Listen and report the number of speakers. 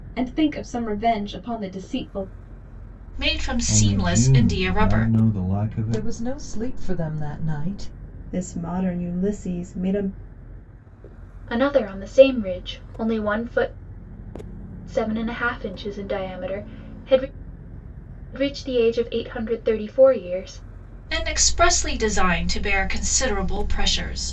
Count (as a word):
six